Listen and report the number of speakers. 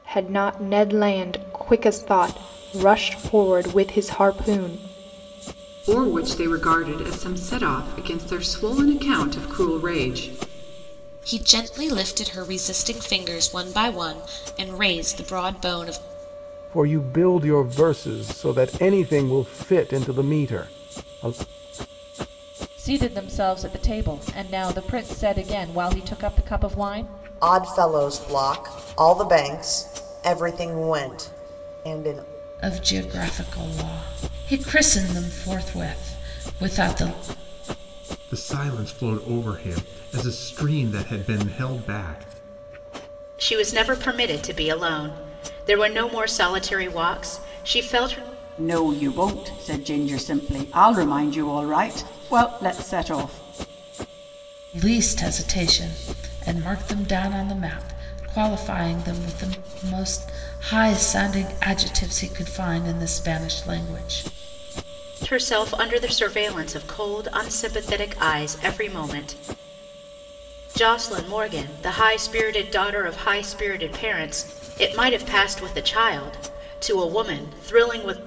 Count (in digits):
10